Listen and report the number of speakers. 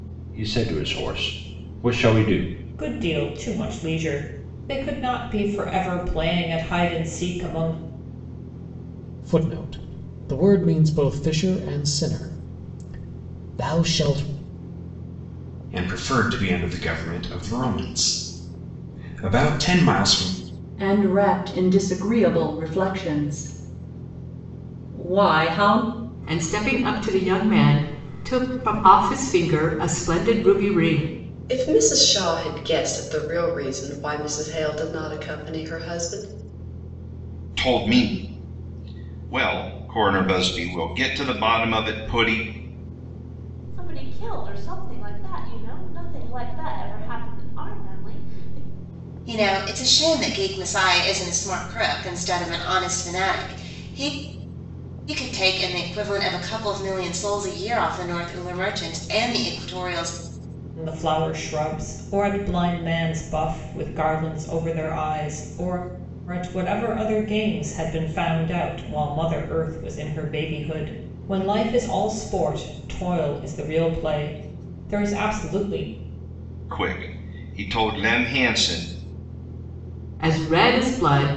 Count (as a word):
ten